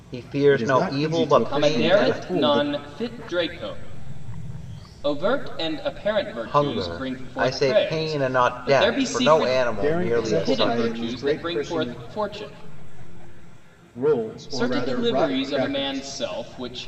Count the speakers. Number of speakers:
three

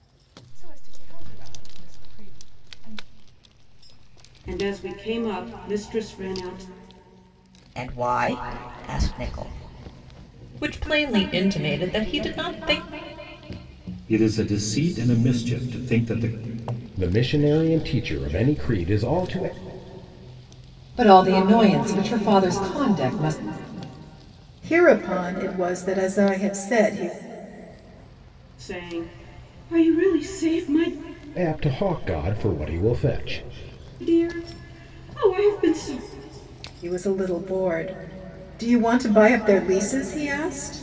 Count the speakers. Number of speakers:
eight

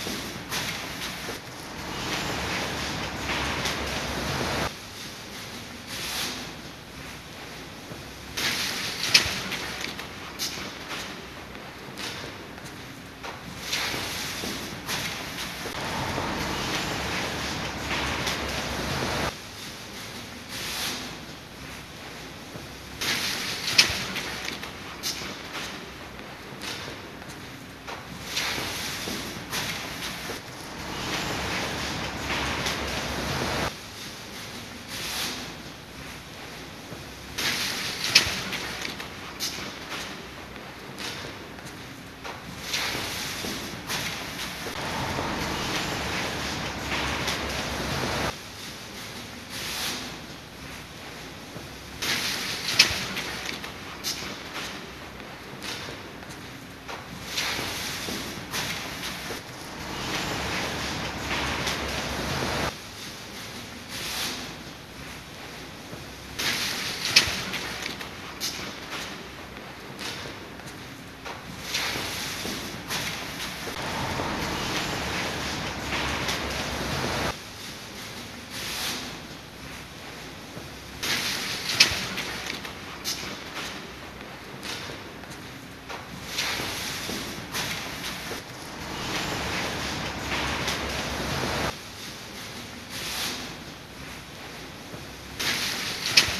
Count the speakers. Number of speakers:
zero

